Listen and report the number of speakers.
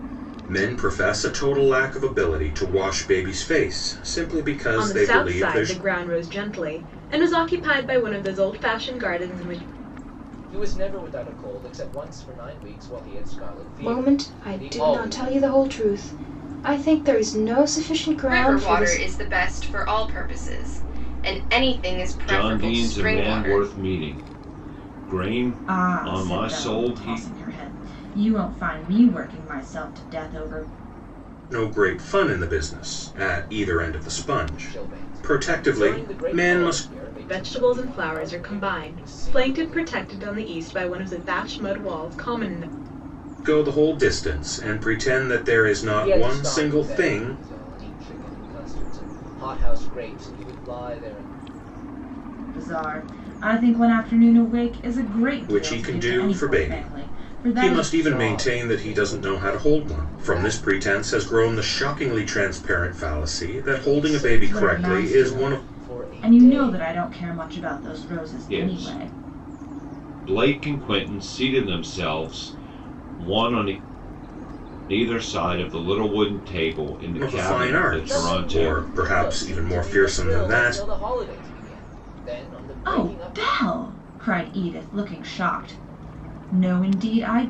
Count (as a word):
seven